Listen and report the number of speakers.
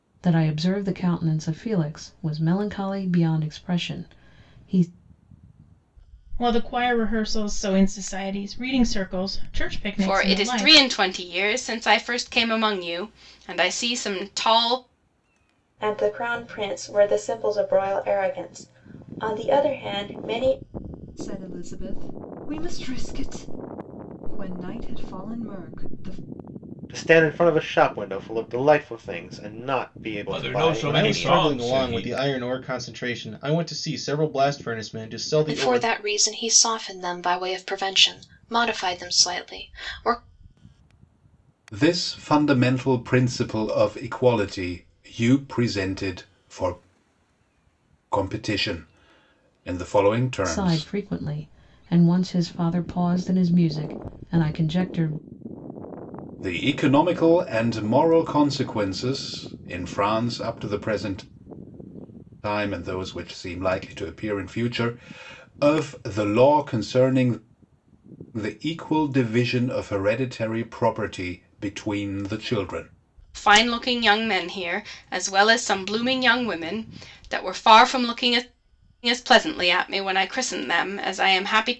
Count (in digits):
10